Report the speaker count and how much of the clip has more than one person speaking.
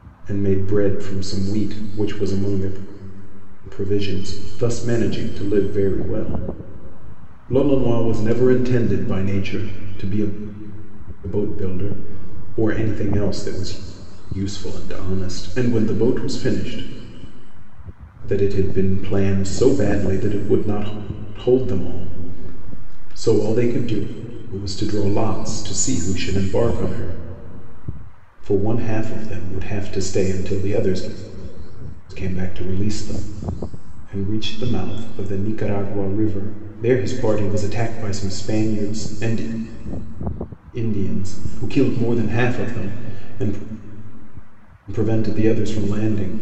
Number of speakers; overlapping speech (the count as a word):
one, no overlap